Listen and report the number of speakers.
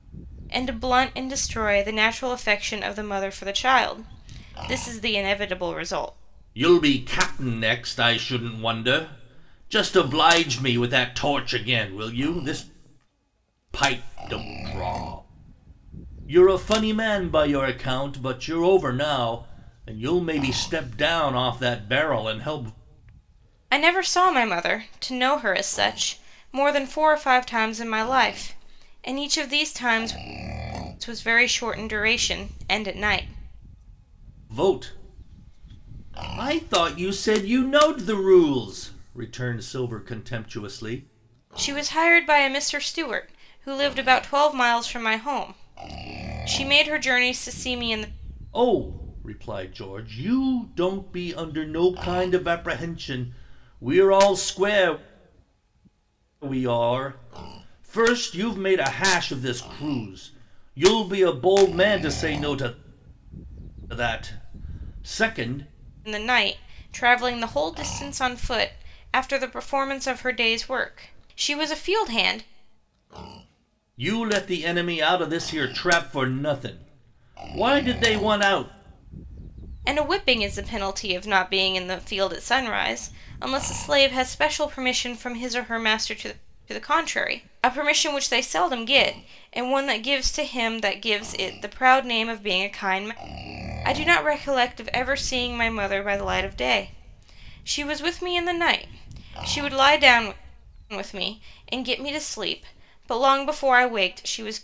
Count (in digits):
2